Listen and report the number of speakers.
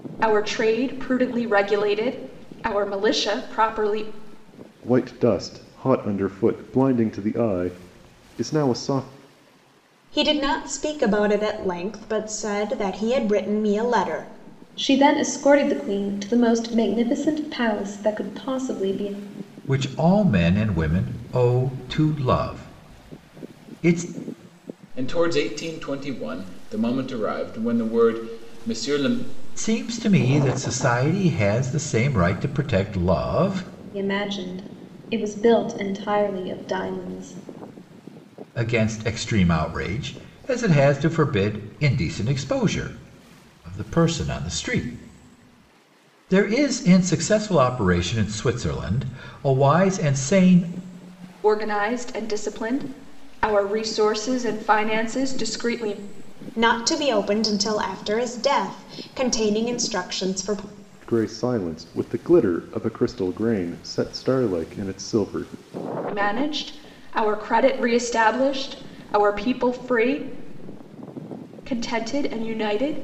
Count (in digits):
6